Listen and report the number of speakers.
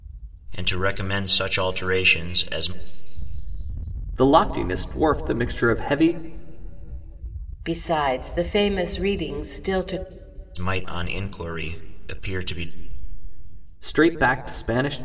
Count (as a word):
three